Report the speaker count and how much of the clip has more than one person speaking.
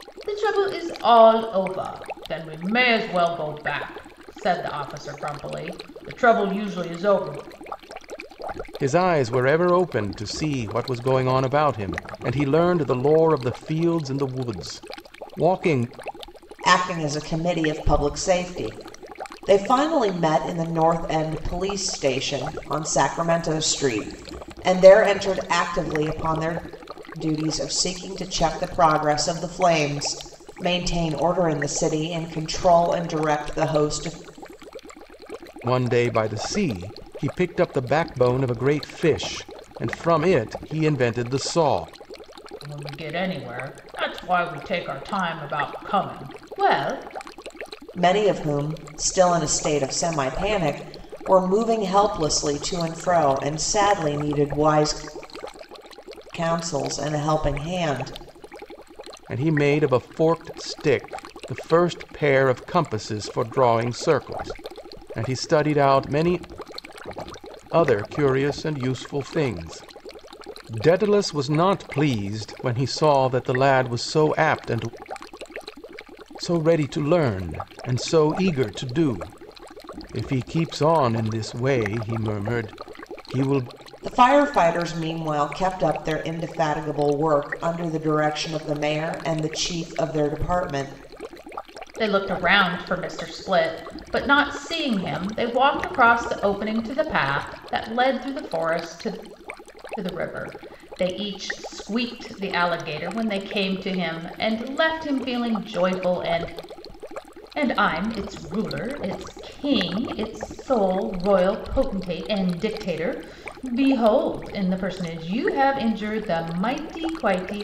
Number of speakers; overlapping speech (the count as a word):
three, no overlap